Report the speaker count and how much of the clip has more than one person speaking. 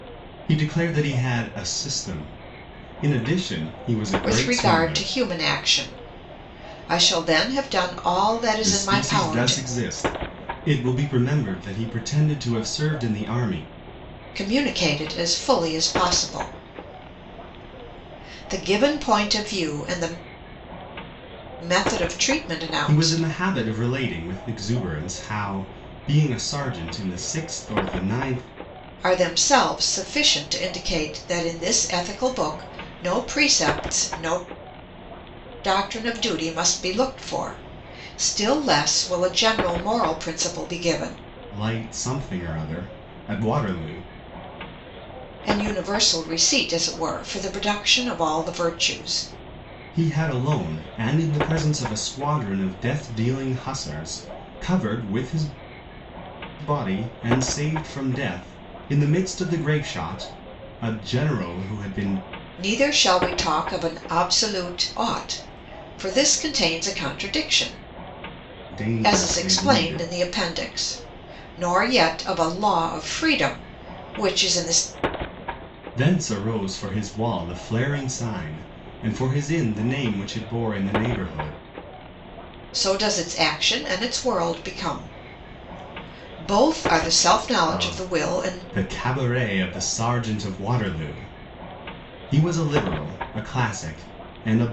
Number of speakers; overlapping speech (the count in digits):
2, about 5%